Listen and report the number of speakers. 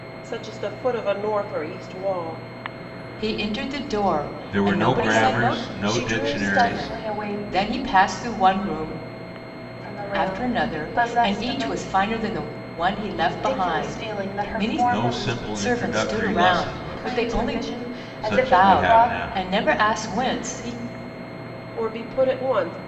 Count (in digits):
4